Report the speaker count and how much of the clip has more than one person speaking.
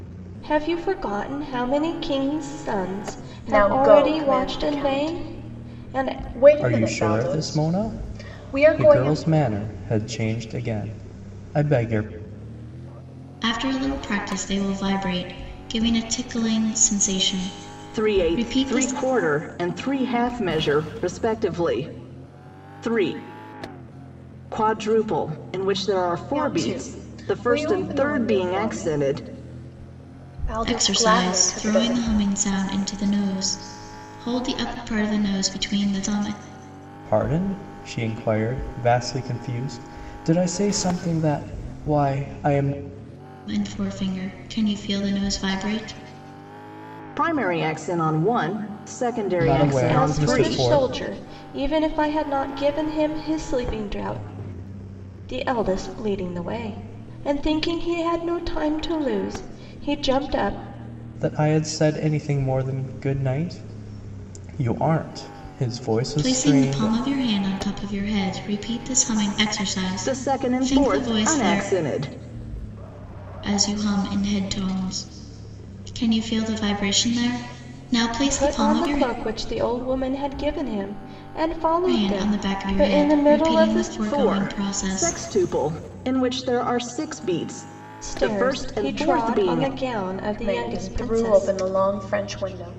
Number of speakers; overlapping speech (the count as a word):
five, about 24%